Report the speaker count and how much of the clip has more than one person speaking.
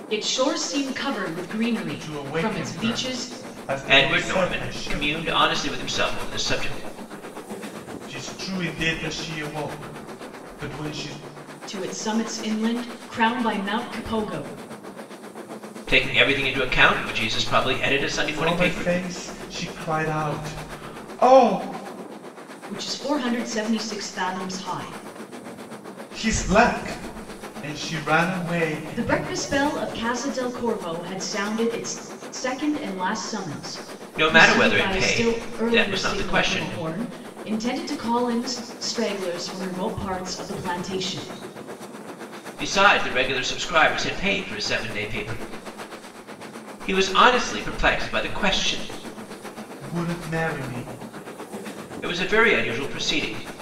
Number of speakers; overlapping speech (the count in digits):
3, about 12%